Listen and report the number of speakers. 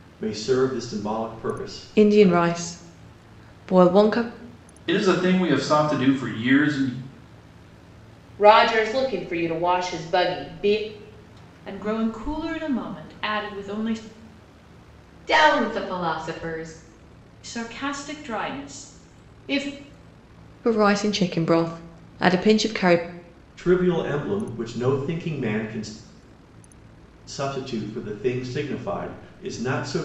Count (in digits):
6